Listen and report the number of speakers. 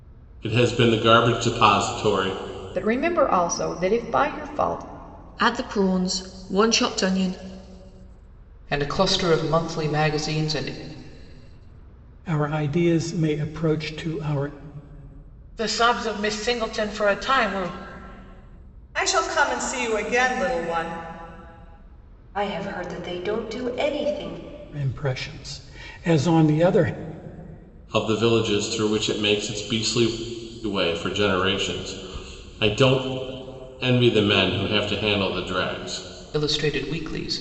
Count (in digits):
8